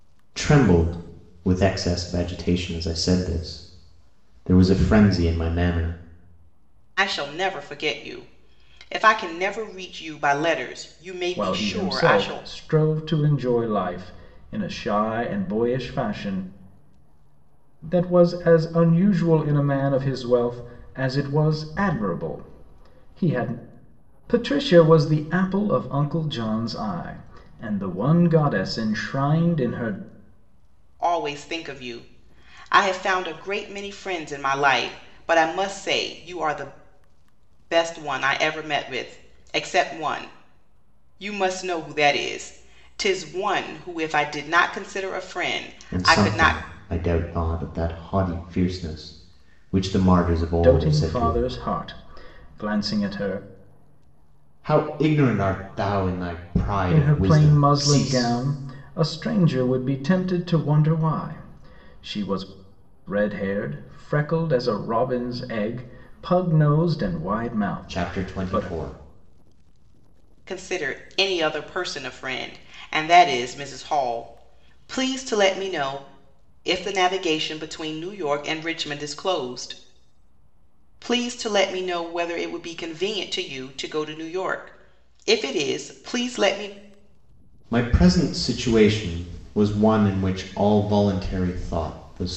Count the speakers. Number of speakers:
3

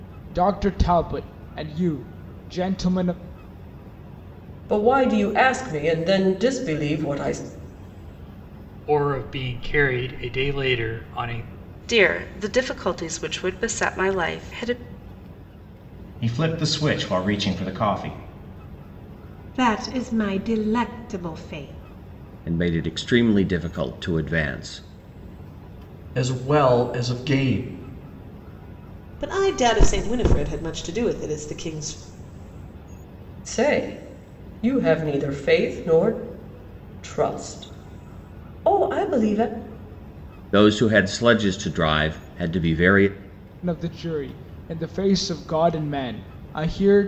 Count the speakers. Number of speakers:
9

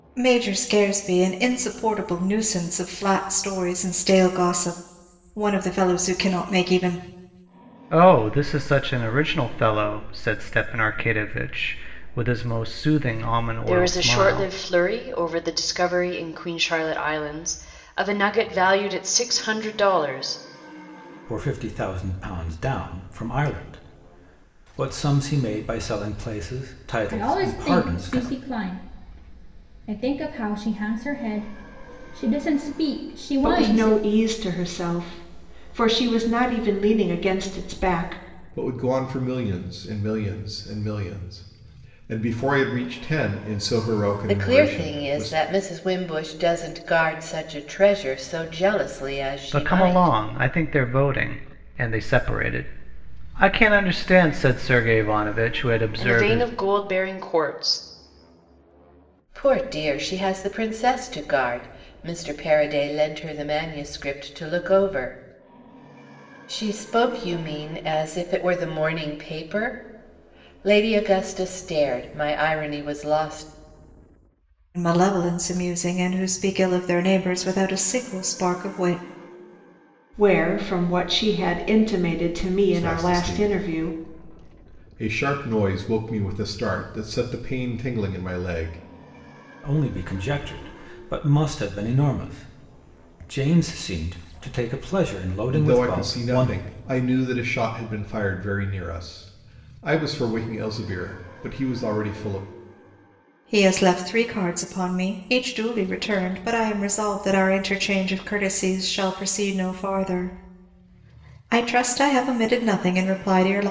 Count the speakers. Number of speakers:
8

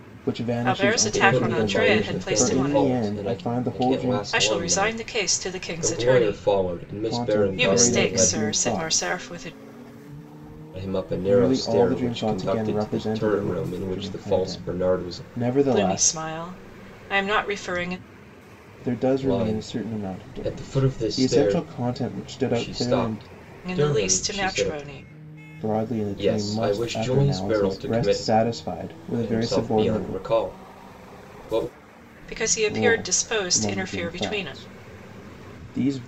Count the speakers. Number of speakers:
3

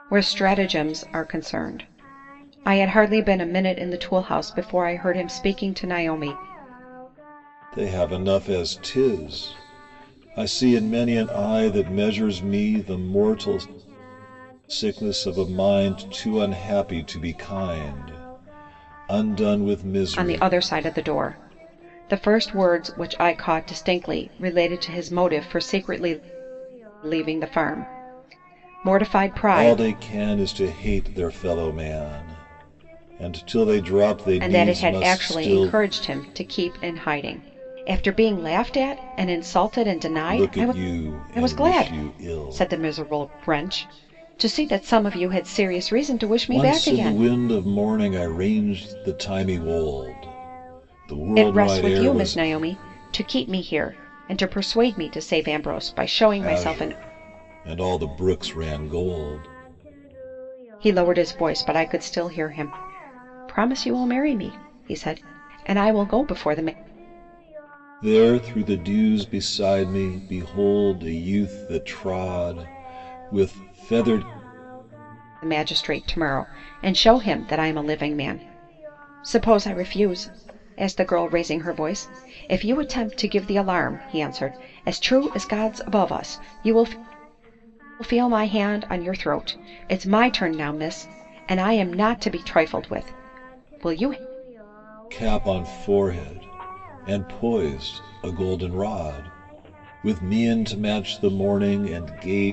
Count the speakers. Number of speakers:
2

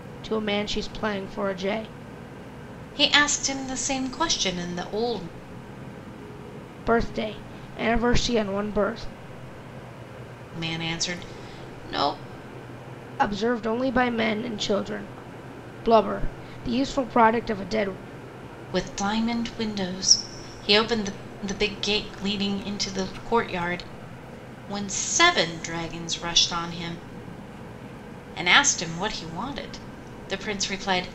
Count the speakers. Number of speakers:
2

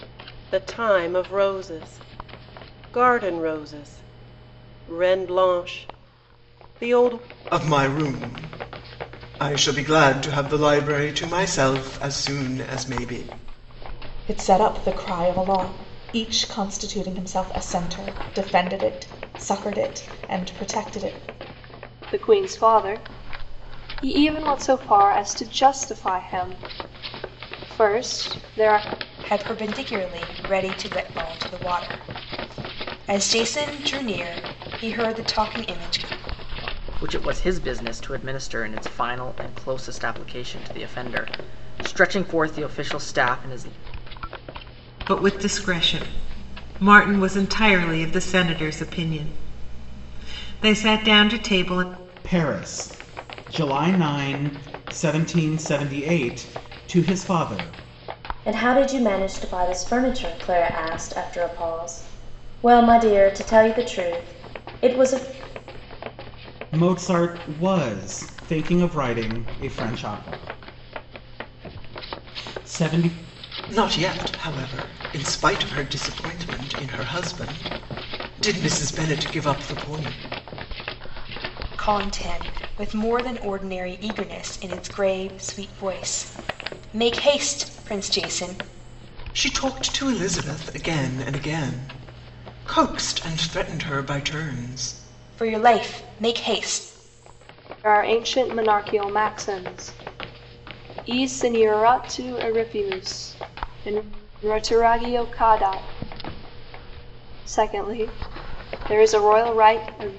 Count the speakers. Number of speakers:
9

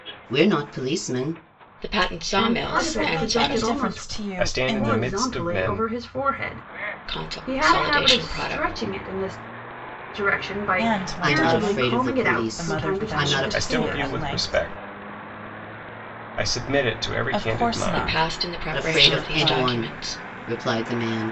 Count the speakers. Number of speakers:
5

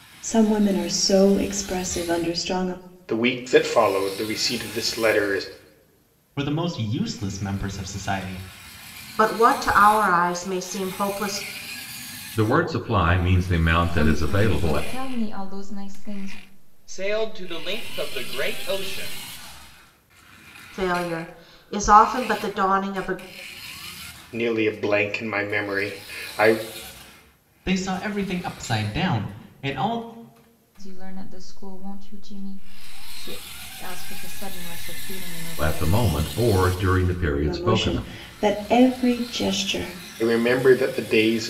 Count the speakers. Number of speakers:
7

